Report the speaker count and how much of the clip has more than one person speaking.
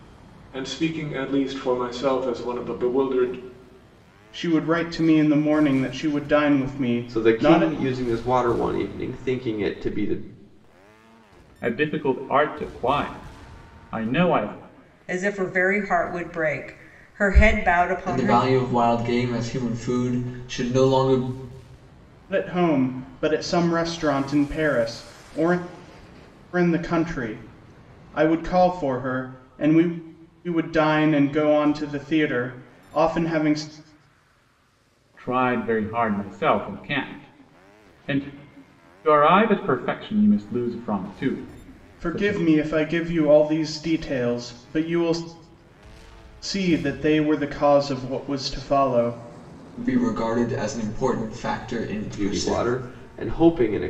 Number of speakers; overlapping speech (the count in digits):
6, about 4%